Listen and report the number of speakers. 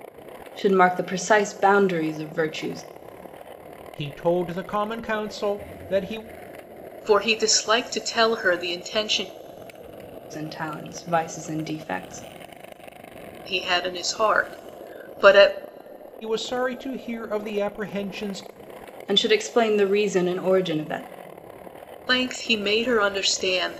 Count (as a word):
three